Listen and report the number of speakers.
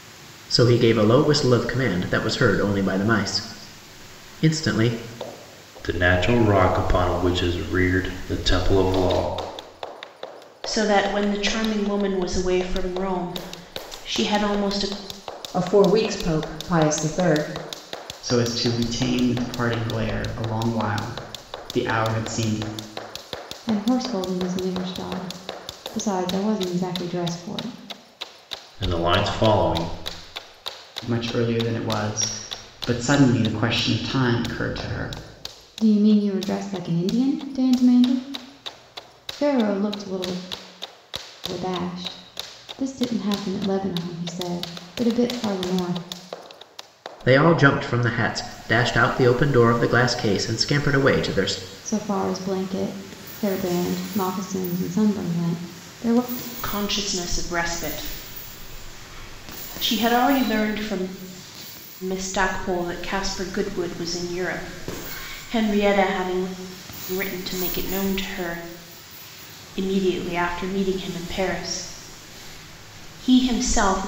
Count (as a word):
six